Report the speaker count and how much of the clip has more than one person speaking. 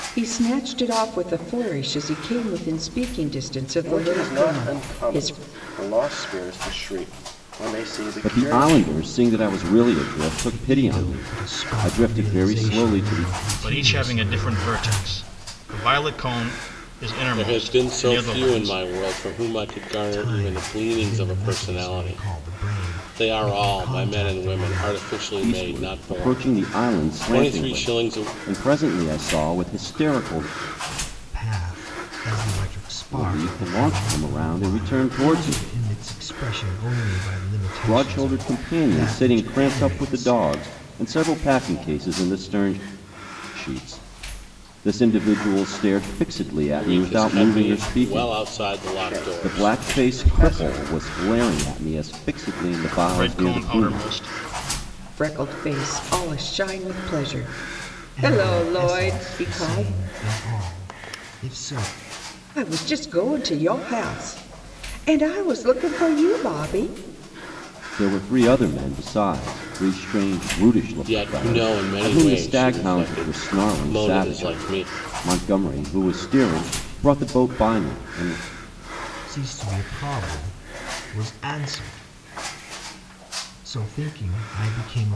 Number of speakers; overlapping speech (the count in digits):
6, about 36%